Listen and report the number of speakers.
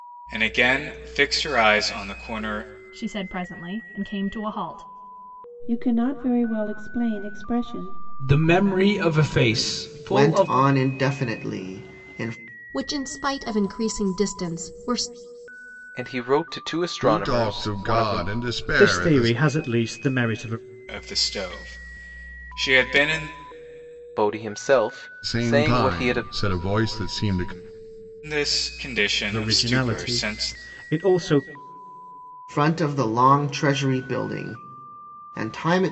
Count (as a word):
nine